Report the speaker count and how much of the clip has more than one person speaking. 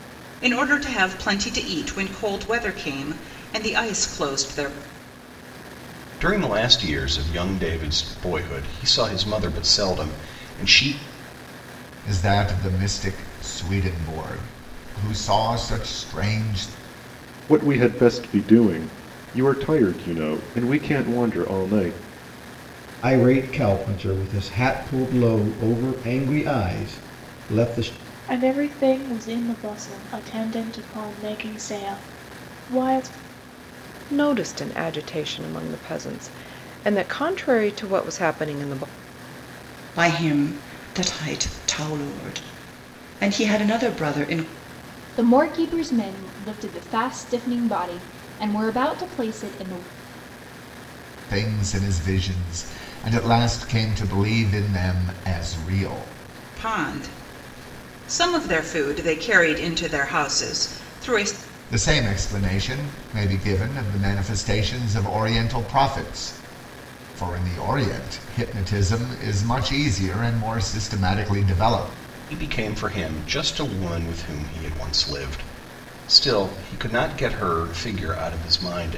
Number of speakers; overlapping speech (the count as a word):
nine, no overlap